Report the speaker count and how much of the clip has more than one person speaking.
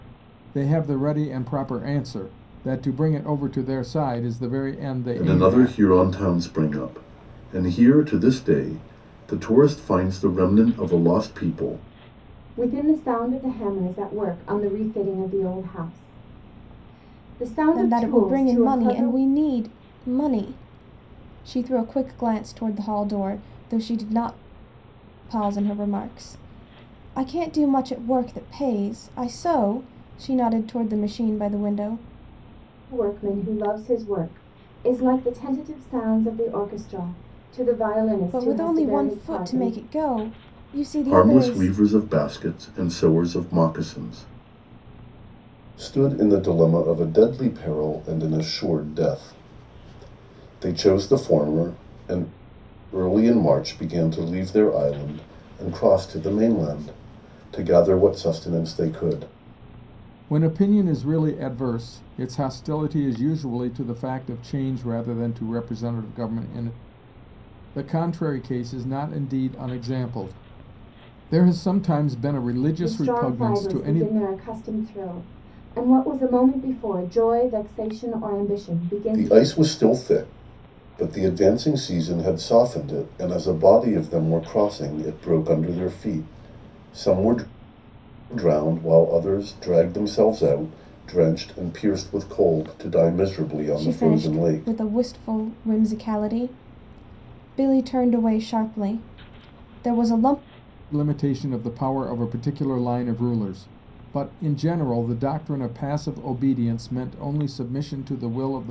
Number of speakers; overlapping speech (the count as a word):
four, about 7%